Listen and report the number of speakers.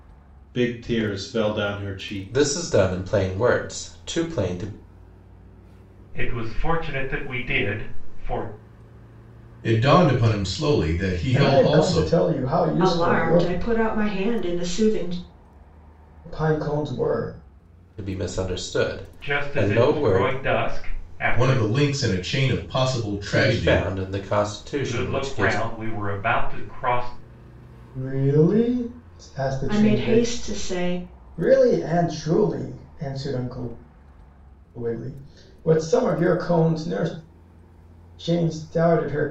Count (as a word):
six